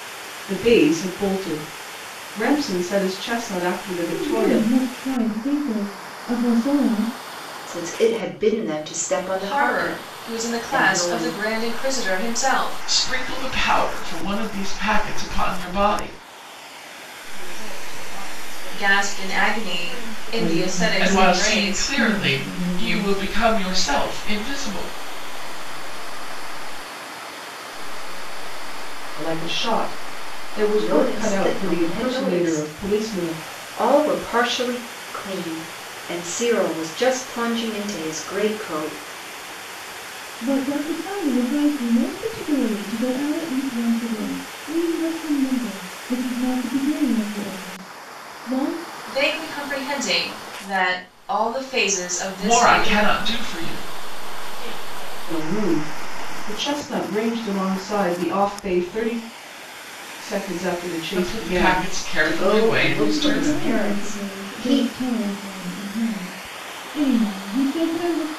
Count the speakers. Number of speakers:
7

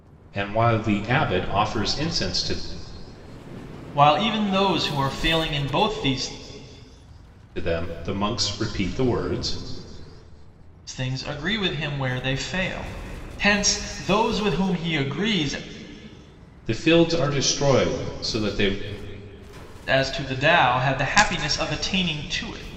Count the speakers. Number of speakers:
2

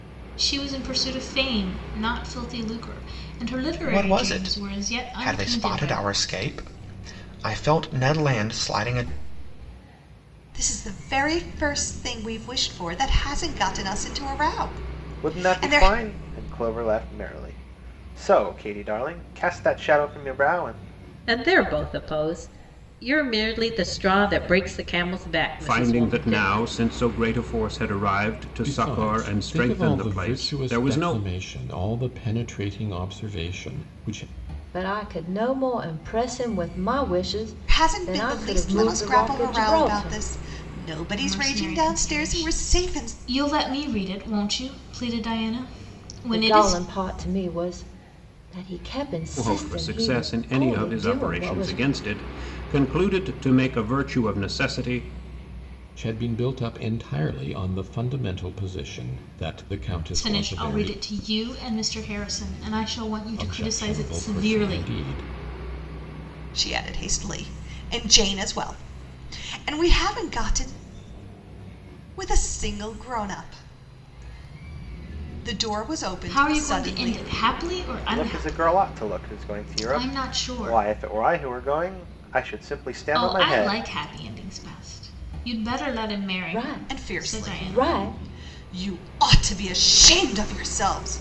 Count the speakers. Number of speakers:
8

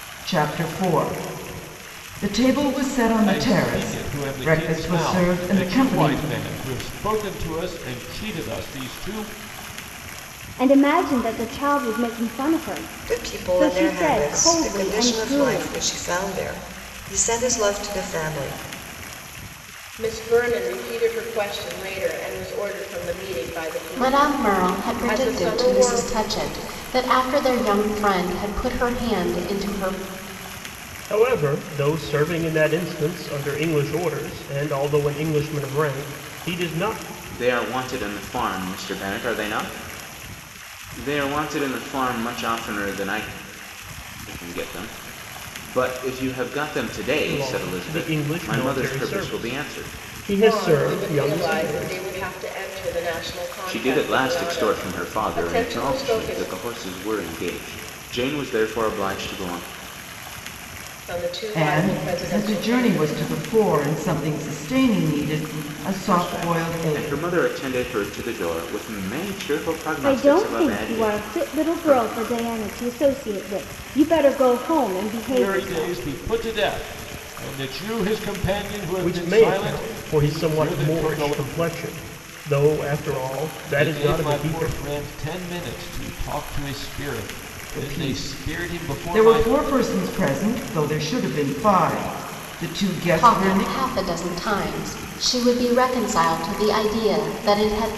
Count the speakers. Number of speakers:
8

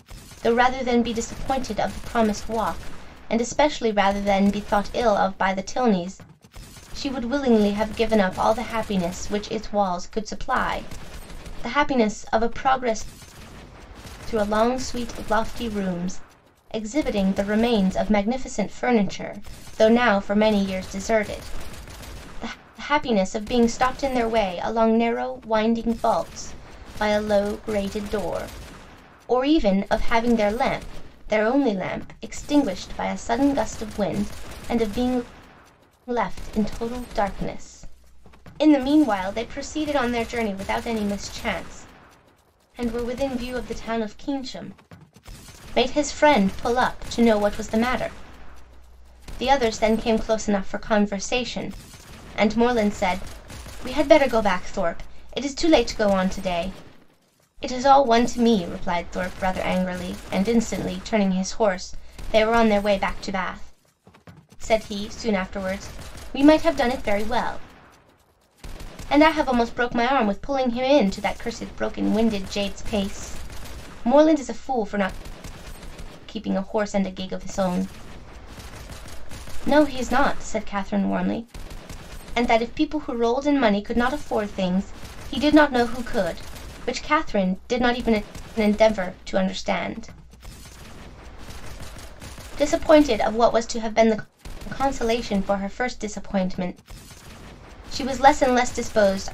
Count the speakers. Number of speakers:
1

